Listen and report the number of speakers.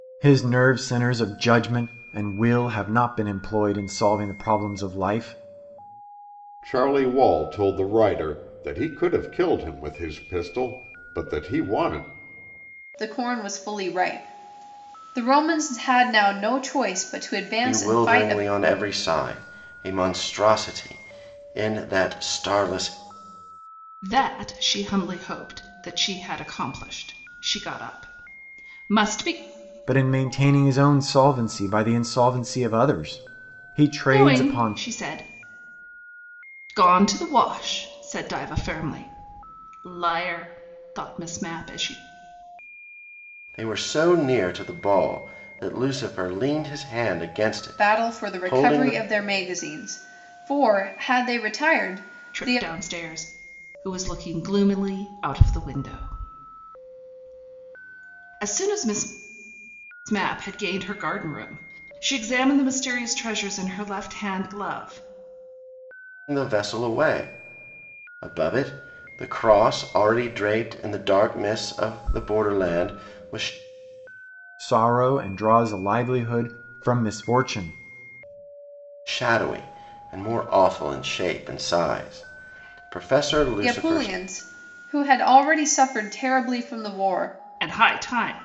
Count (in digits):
5